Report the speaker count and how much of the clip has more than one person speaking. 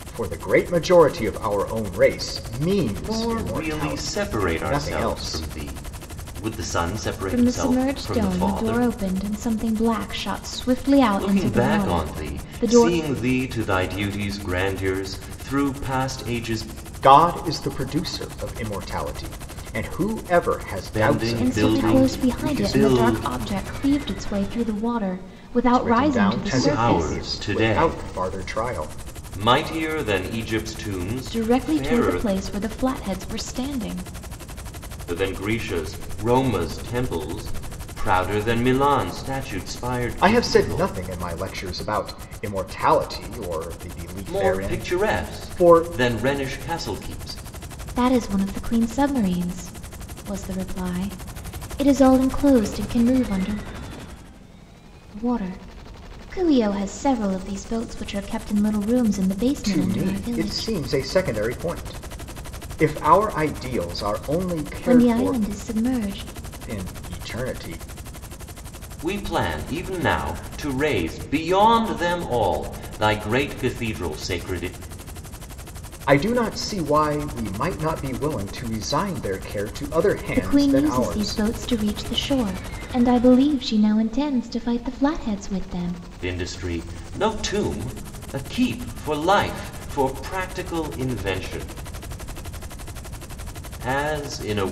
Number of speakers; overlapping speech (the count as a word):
three, about 19%